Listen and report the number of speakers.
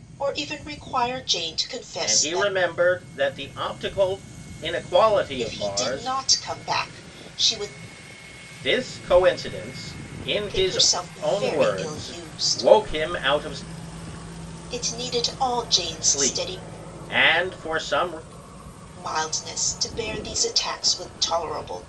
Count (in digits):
2